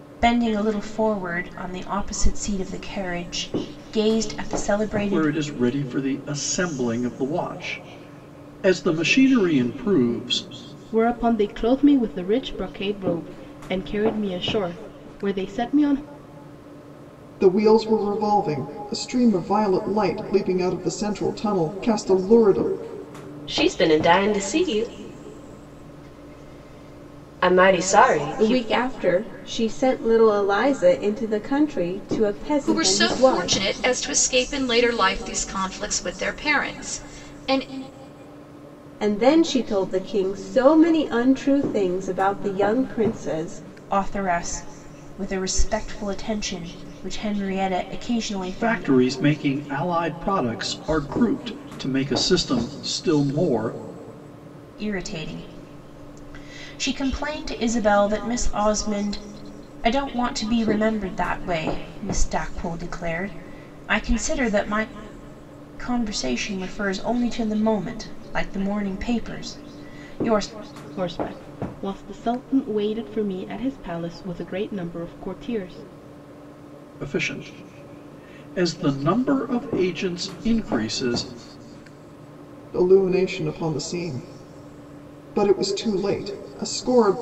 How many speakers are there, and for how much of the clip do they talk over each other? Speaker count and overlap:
7, about 3%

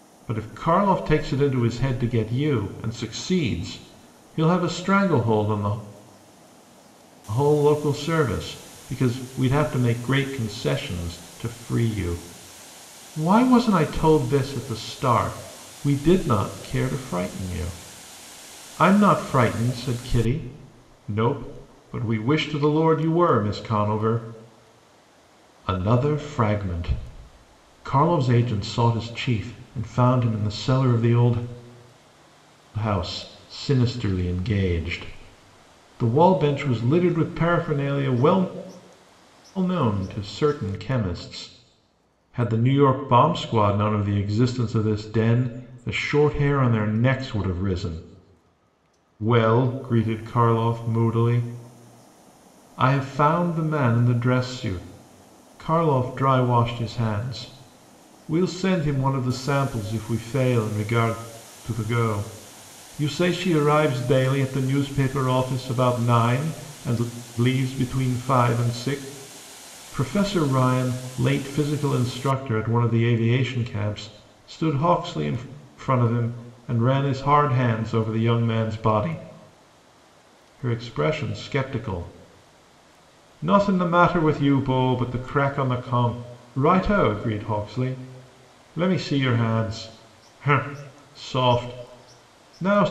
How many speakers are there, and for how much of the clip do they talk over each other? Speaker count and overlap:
1, no overlap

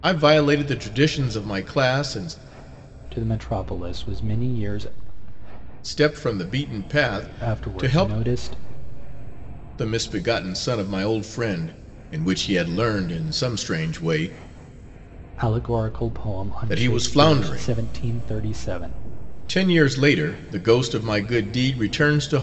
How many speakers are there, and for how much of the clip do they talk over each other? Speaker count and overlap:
2, about 9%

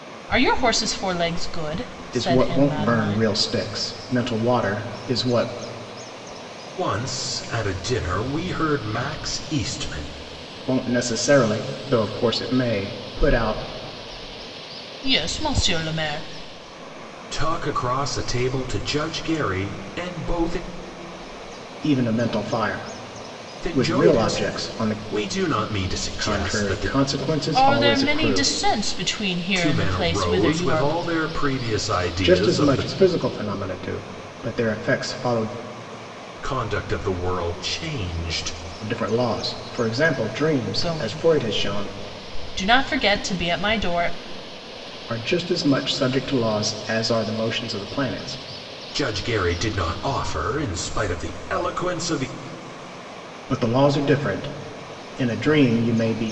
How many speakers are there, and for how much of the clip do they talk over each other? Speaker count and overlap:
3, about 14%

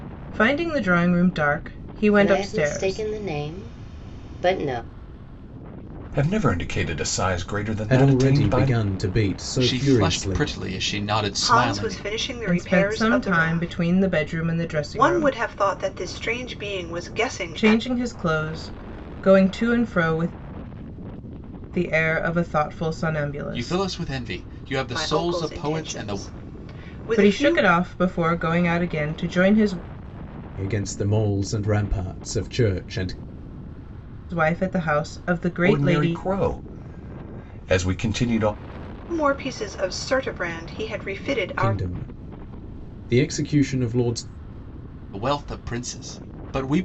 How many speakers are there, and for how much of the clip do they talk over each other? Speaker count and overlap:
6, about 19%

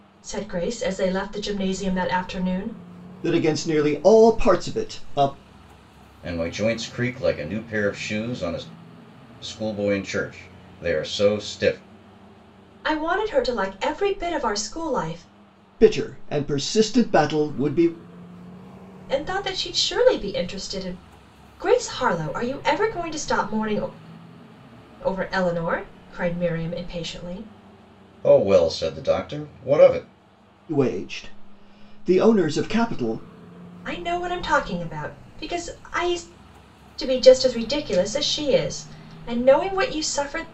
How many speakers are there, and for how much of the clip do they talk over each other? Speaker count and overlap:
3, no overlap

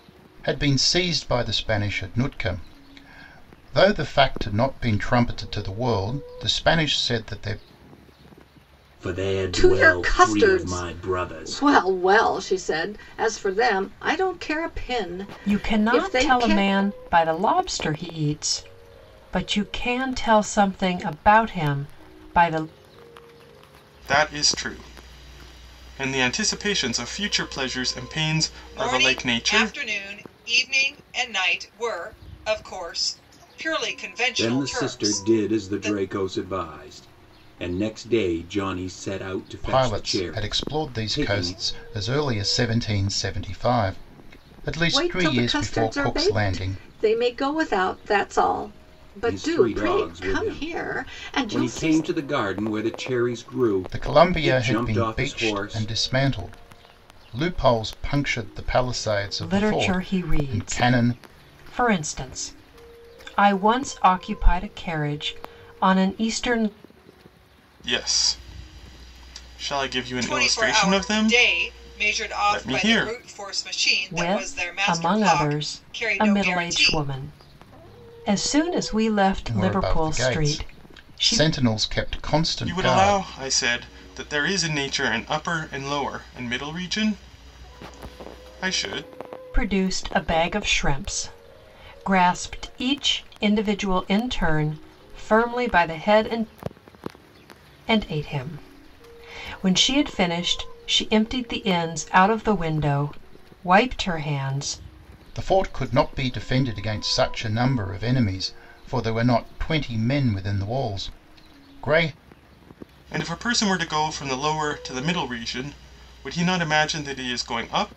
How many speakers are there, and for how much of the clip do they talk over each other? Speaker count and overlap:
6, about 22%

